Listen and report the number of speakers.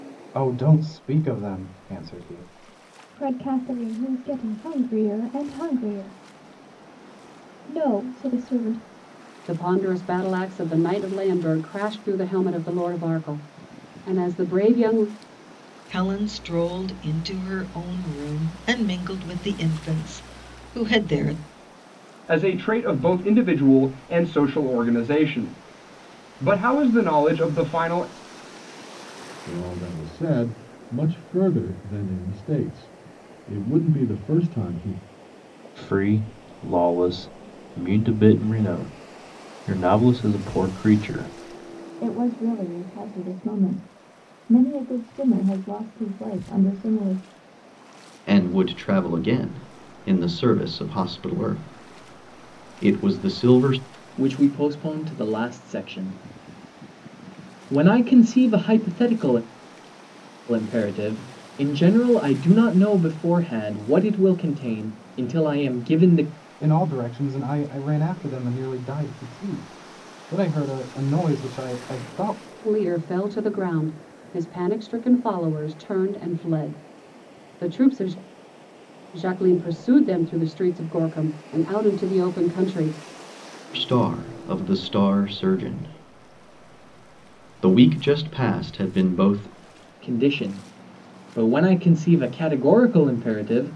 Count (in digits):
10